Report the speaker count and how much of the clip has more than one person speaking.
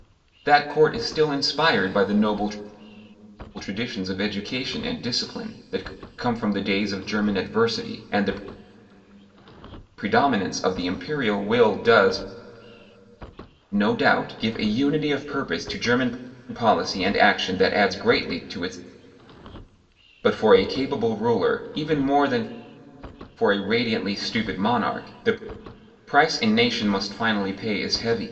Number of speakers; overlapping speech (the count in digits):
1, no overlap